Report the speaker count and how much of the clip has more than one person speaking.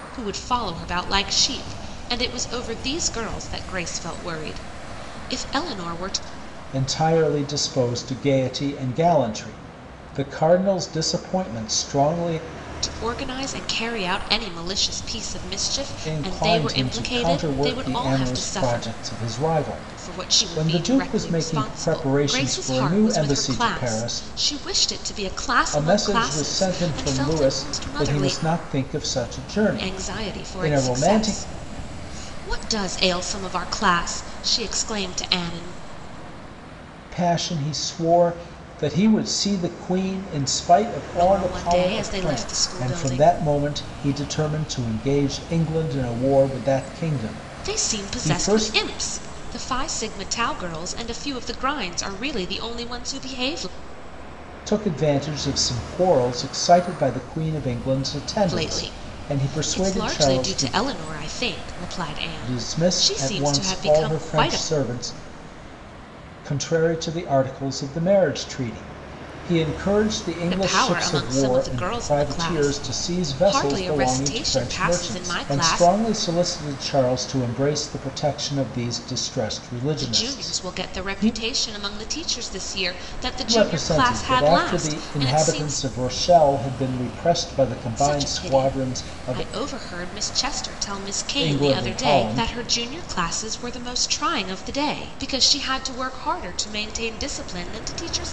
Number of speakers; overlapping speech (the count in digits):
2, about 31%